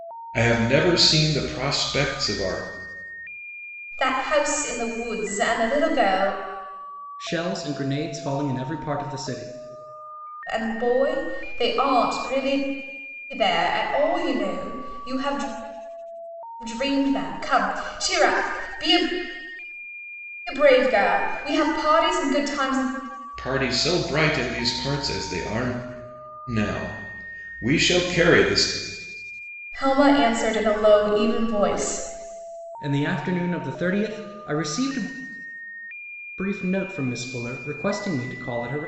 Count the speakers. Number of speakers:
3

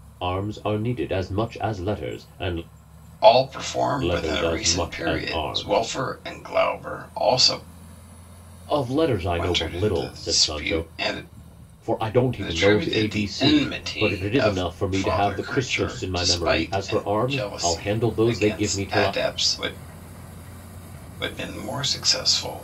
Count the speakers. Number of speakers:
2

